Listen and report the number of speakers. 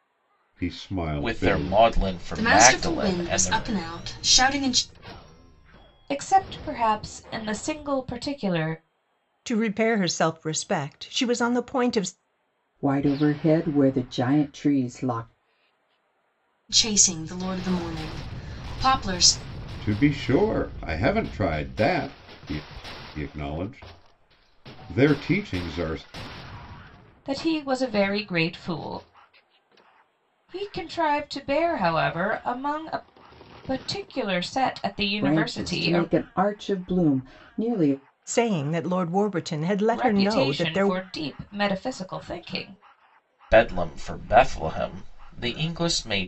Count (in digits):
6